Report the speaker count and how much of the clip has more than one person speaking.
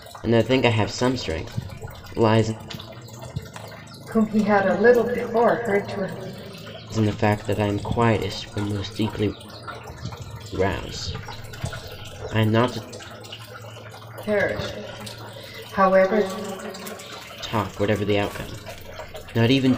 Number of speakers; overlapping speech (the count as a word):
two, no overlap